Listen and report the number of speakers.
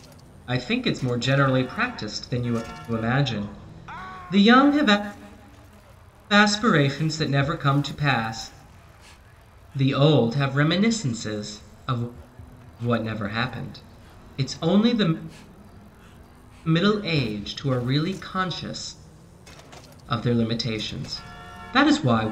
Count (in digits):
1